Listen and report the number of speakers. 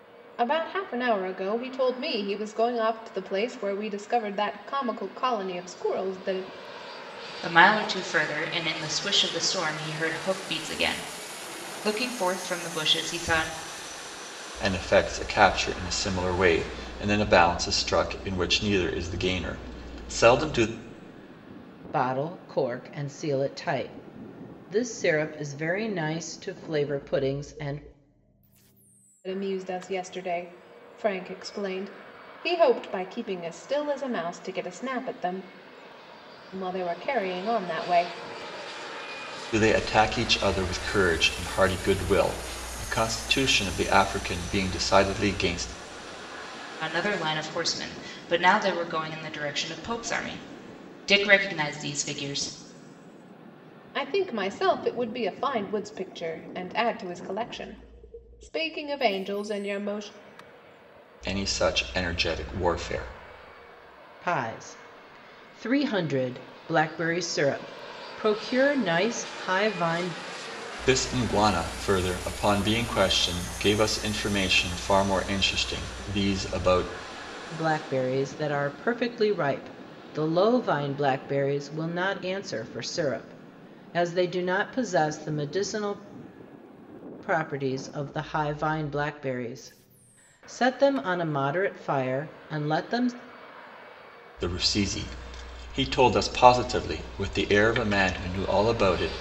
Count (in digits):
4